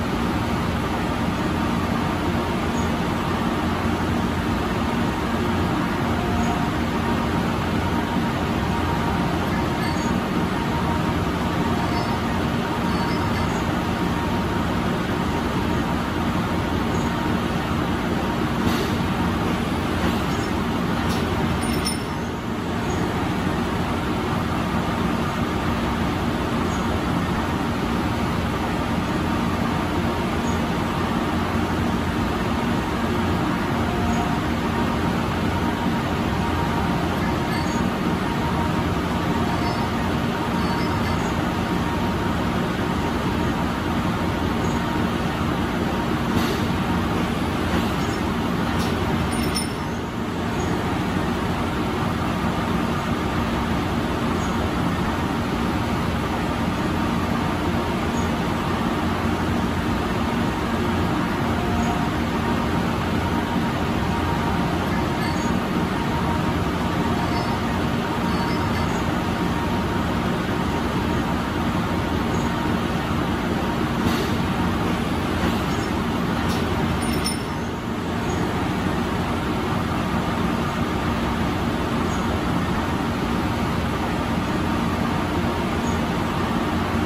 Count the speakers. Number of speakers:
0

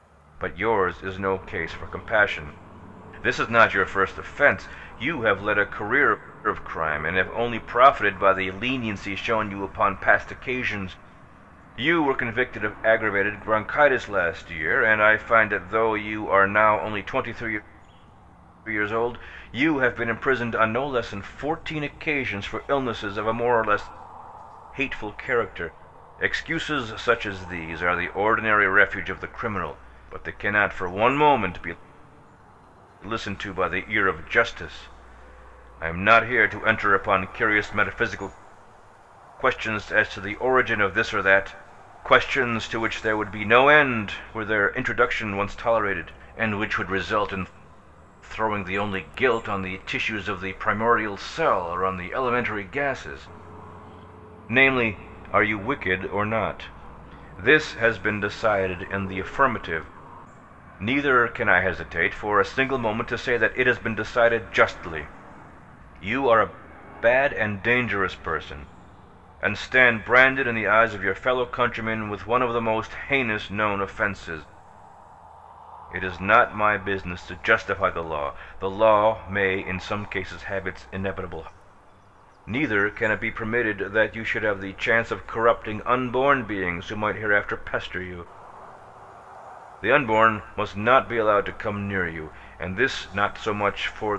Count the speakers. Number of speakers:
1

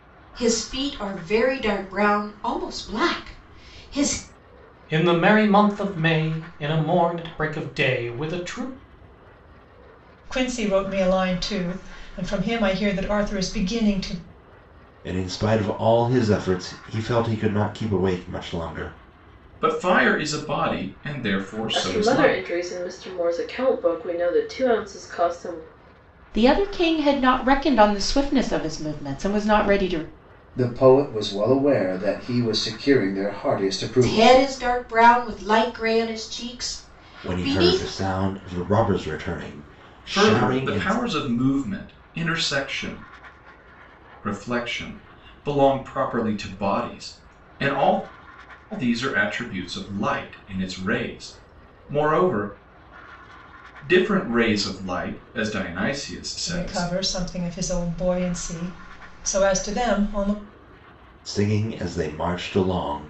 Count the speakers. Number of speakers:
8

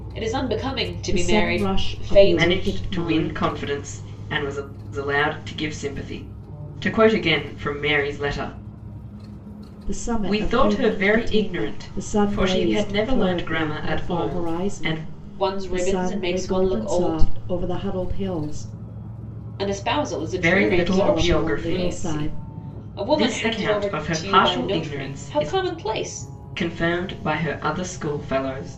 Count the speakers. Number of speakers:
3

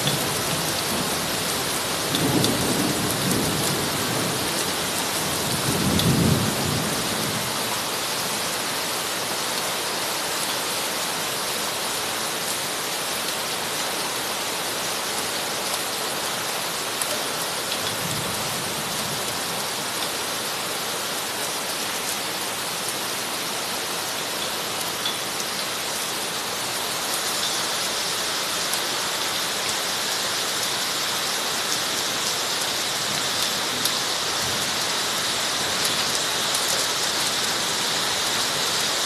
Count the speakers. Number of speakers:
0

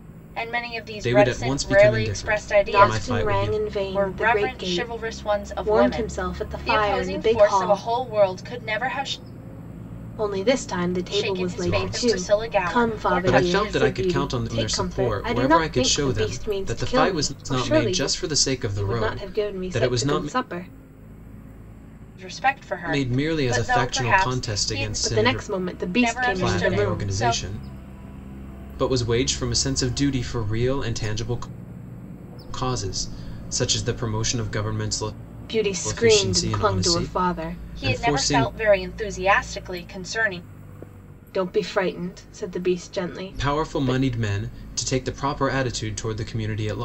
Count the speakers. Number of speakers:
3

